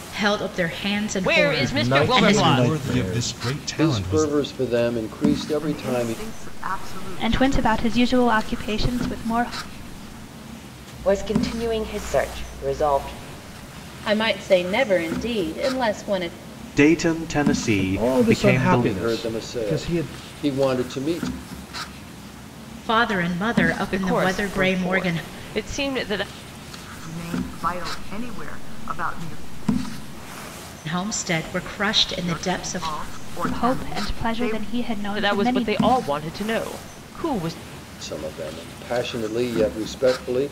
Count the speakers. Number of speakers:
10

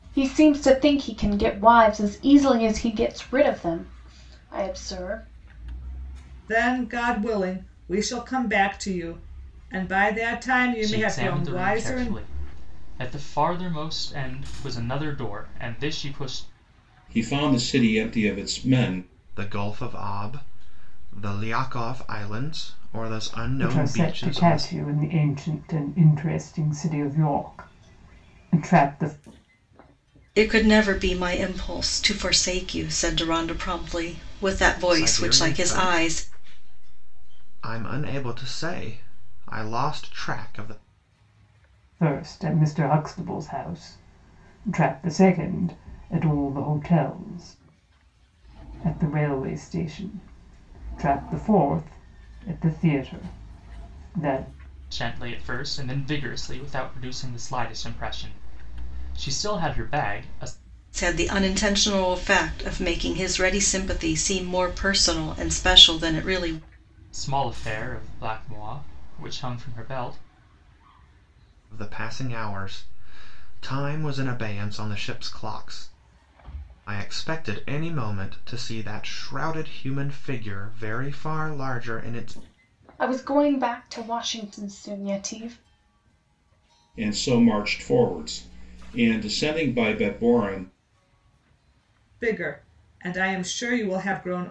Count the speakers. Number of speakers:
7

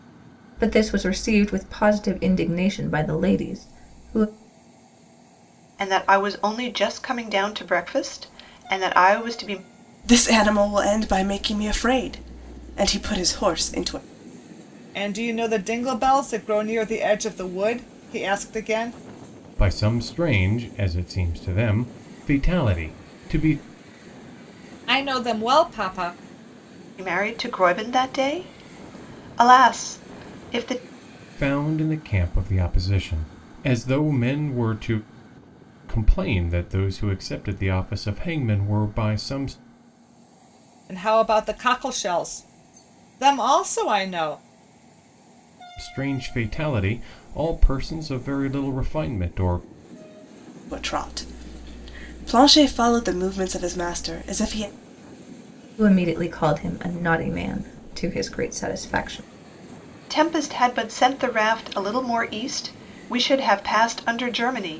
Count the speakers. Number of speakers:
5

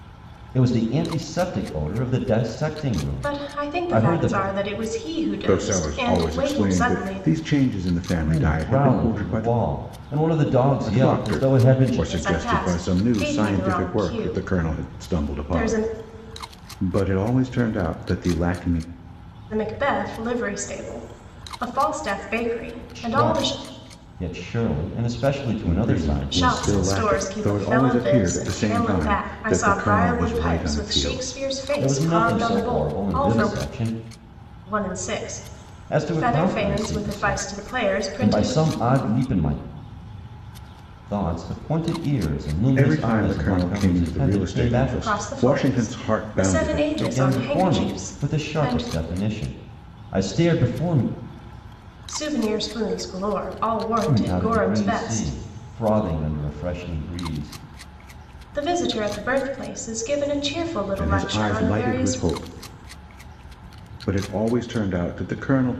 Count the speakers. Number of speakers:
3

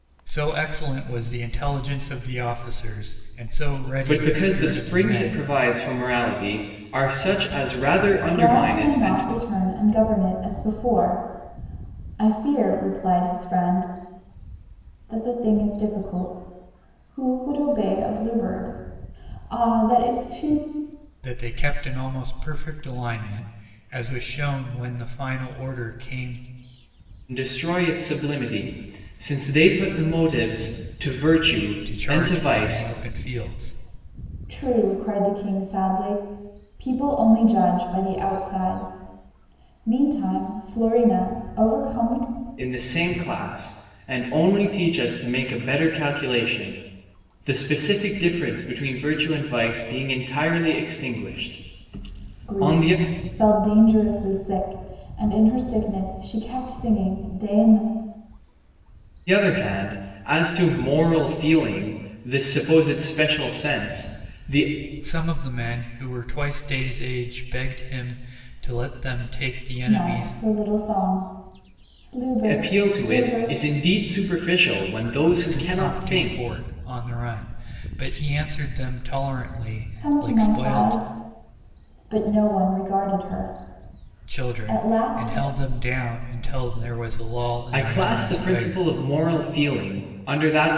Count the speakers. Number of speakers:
3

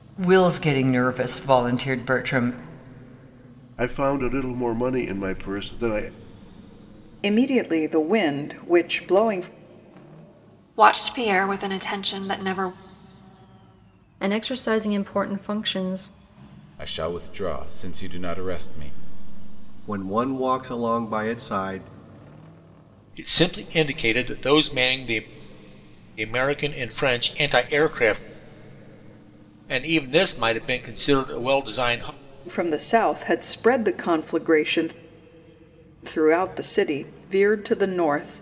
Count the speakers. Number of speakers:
8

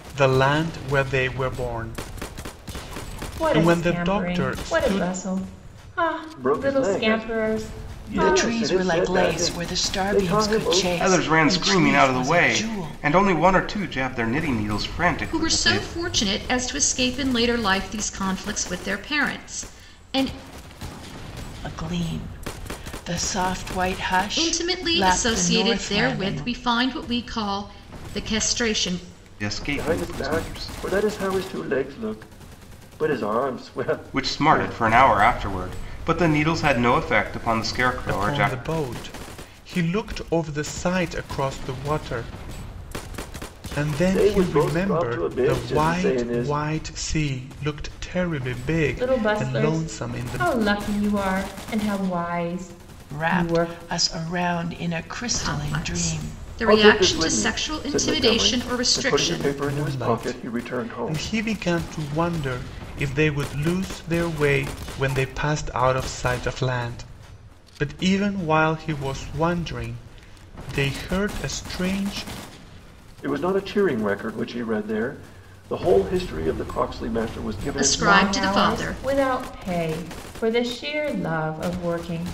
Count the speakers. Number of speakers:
6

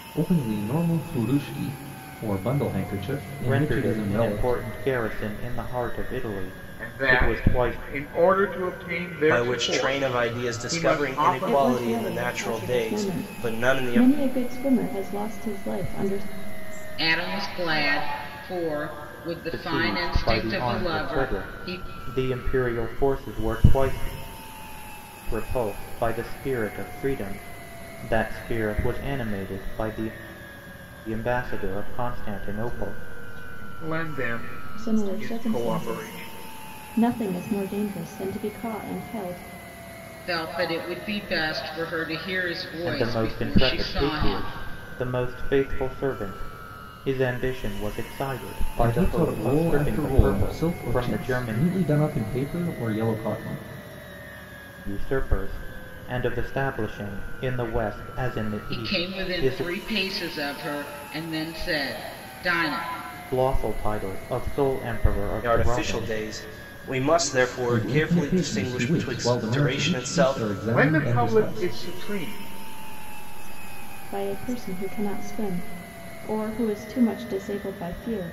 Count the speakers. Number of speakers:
7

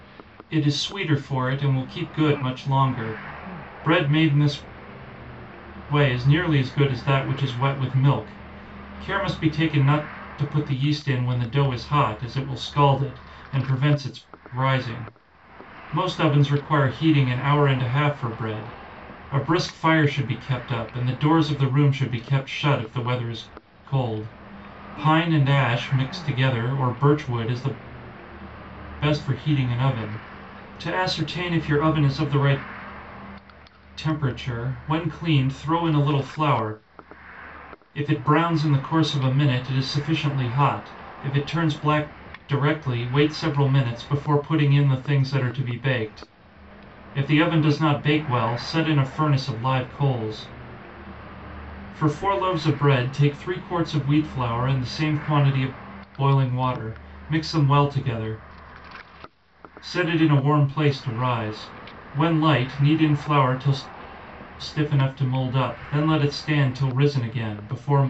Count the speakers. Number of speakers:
1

